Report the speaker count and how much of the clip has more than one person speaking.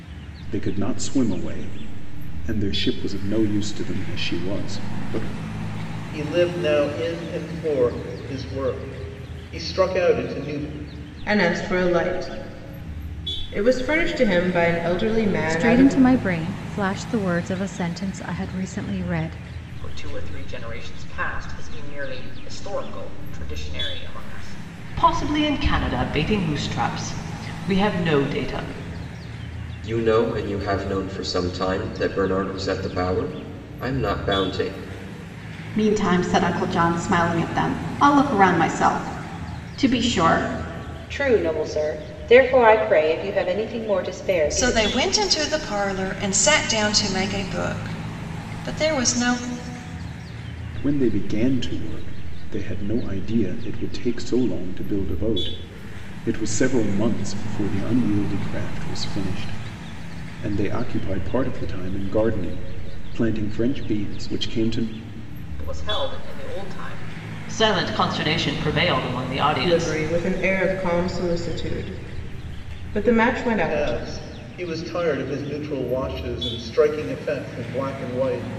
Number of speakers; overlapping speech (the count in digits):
10, about 2%